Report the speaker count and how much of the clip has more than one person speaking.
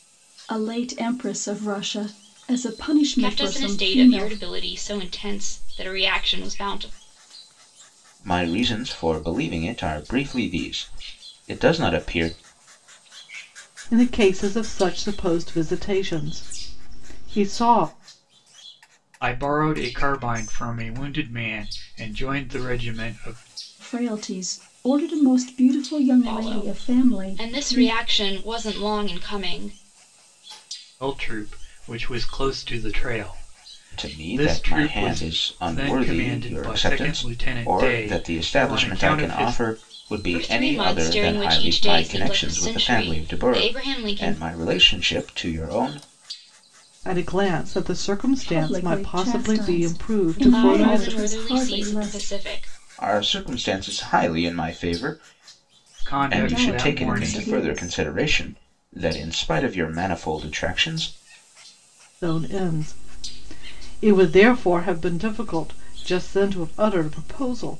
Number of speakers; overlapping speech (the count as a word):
five, about 26%